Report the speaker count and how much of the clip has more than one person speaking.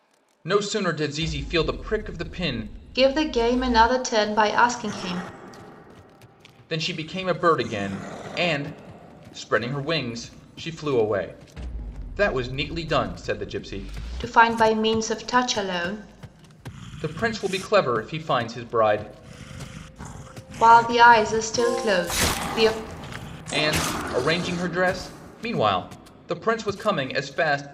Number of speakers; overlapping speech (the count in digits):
2, no overlap